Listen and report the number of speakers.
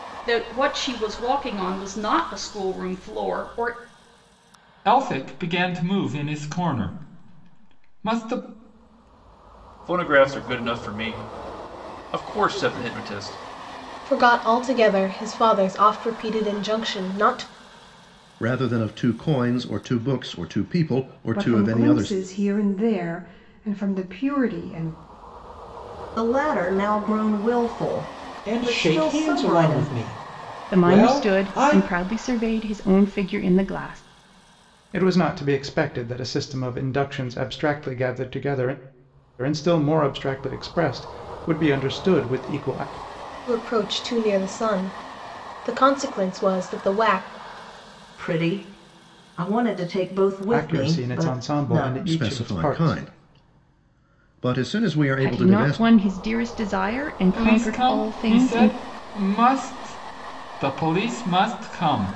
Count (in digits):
10